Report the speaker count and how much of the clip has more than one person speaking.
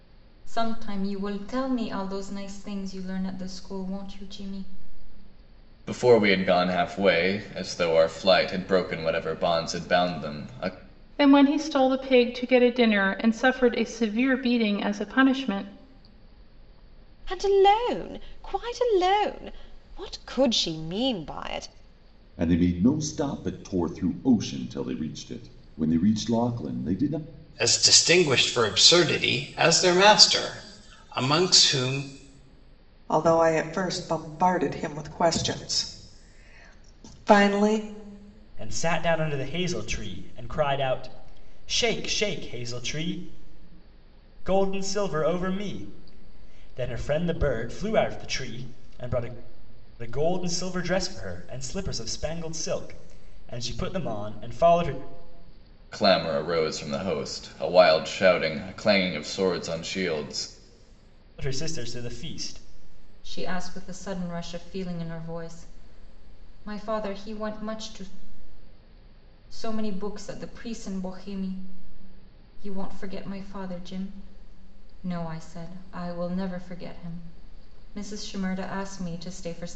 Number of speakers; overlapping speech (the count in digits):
8, no overlap